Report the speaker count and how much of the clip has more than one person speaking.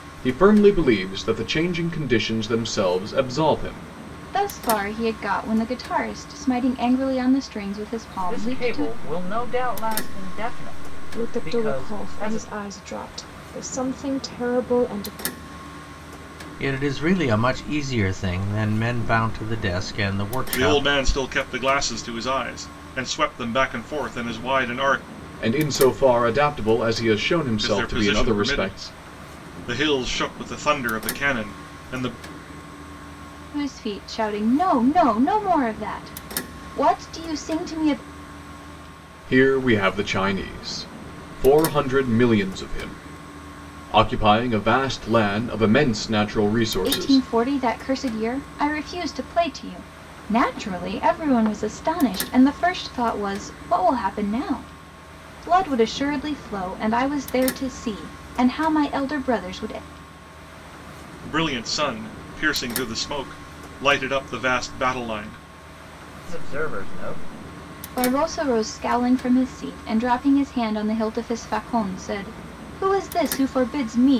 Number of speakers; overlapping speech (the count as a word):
six, about 6%